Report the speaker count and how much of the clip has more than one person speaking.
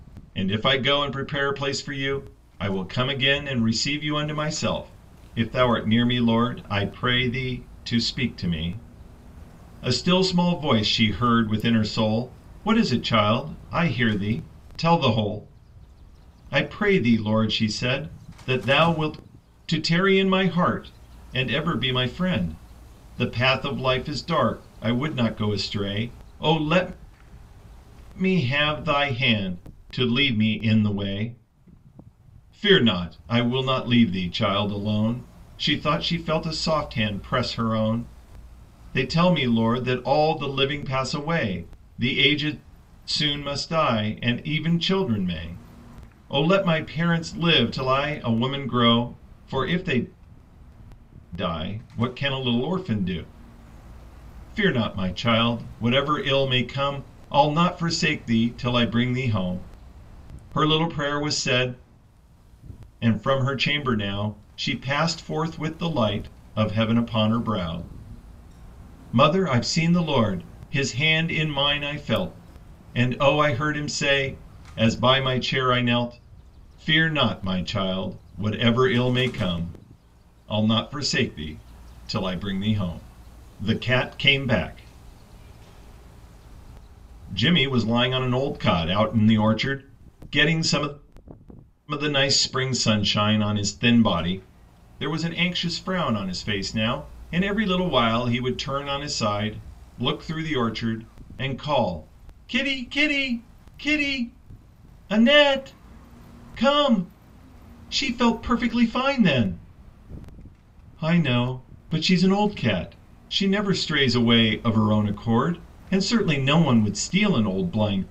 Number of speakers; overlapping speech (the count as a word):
one, no overlap